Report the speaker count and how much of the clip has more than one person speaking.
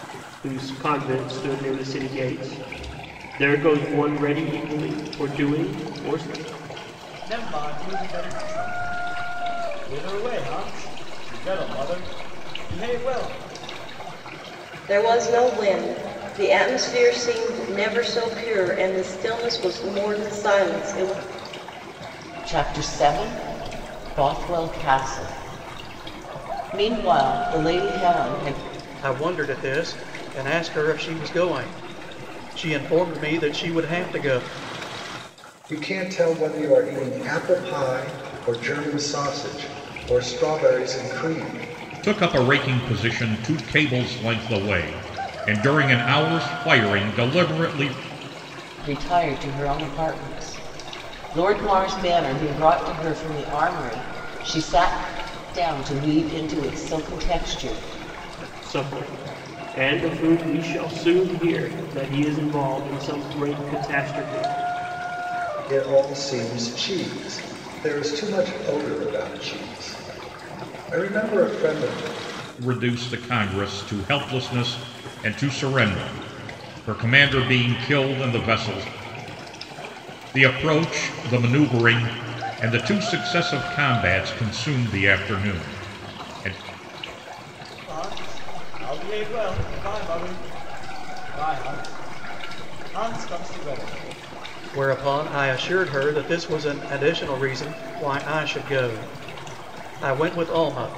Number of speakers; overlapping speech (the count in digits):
7, no overlap